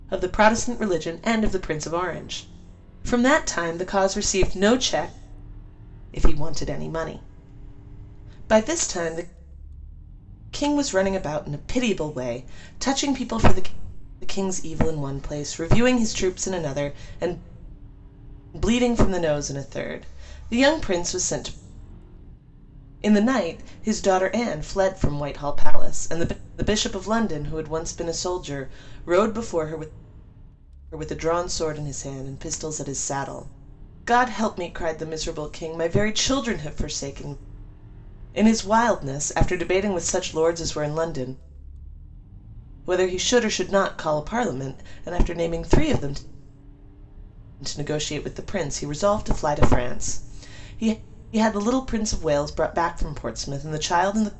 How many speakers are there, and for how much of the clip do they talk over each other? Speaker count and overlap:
1, no overlap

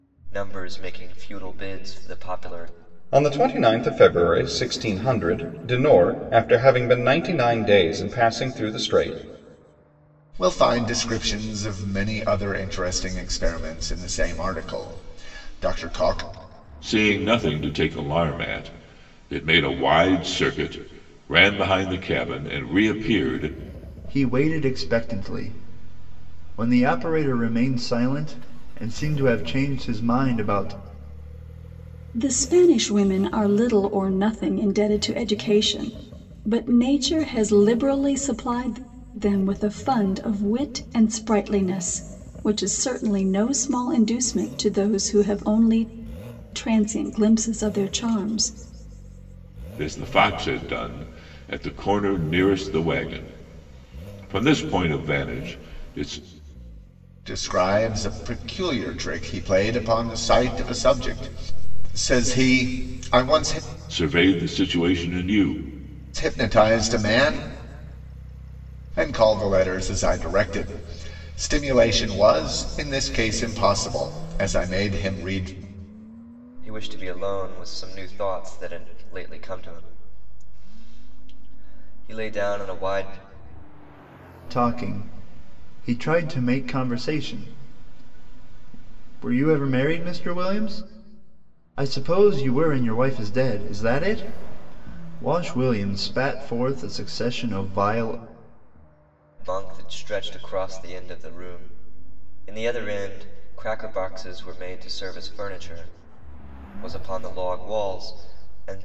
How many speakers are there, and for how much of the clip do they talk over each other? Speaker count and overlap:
6, no overlap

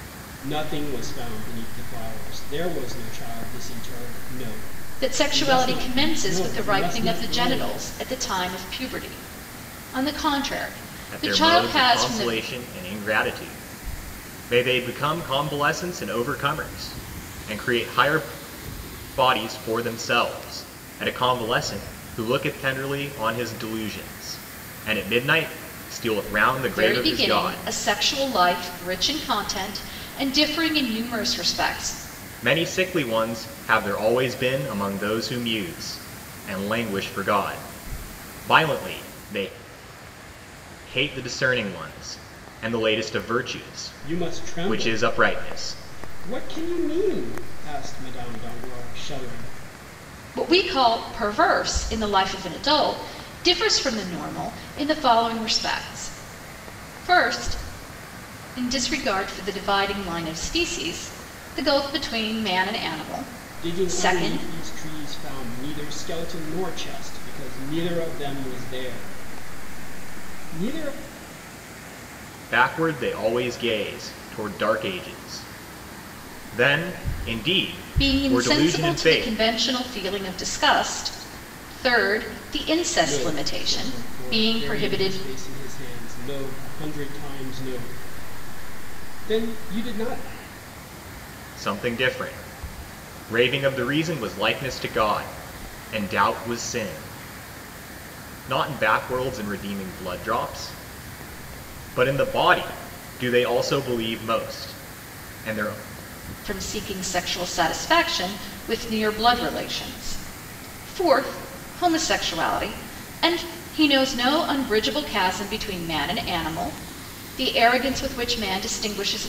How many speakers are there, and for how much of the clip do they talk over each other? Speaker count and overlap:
3, about 10%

